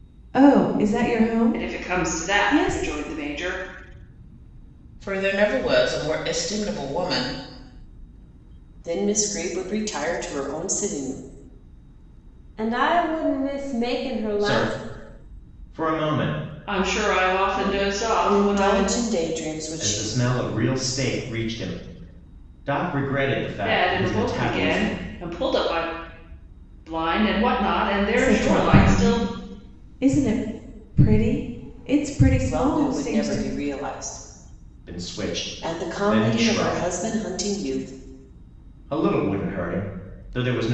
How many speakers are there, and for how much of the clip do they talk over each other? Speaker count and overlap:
6, about 21%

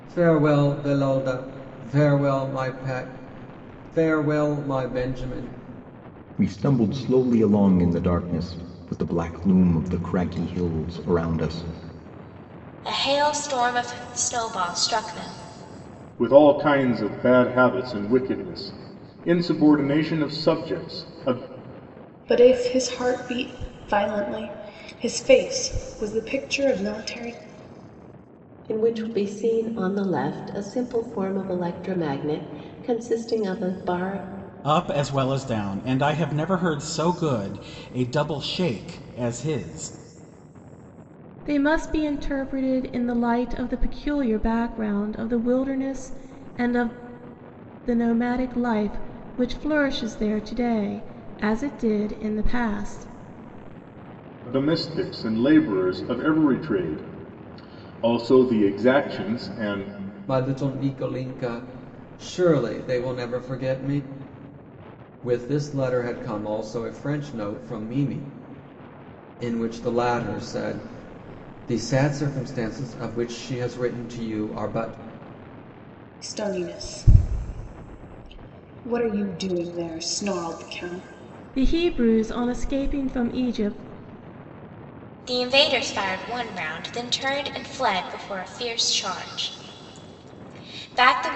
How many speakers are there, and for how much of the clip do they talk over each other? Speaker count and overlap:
8, no overlap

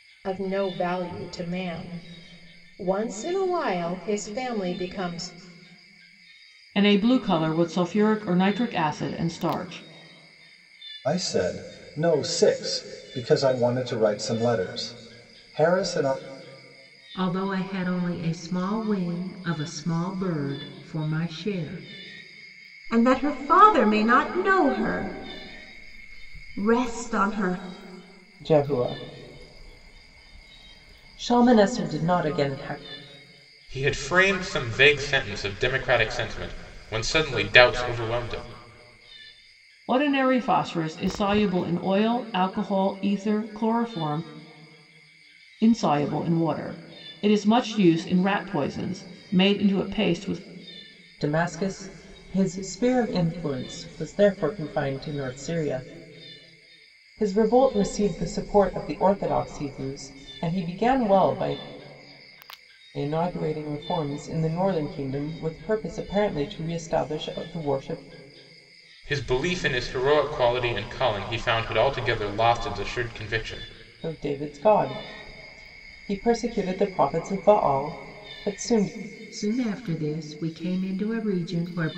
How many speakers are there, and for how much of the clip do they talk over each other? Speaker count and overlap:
7, no overlap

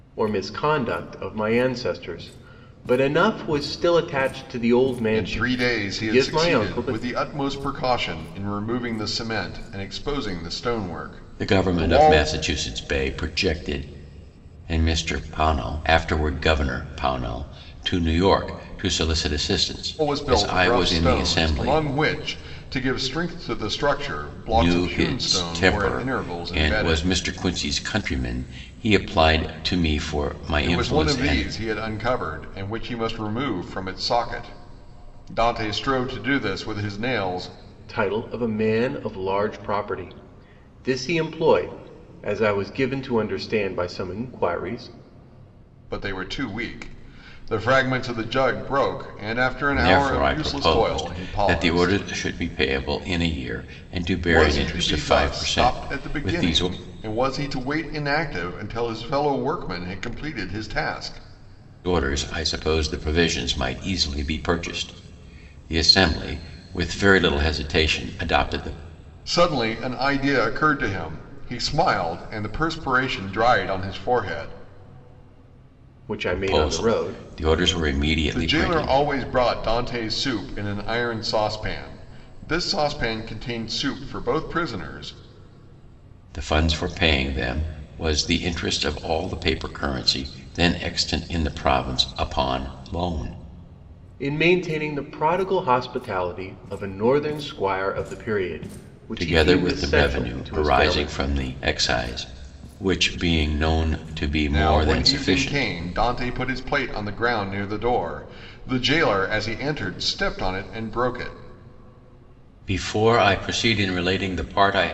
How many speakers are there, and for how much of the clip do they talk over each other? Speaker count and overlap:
3, about 16%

